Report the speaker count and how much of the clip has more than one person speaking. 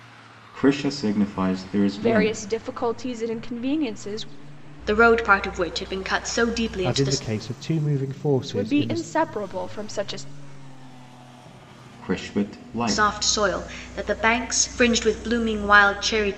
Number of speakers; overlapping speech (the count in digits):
4, about 11%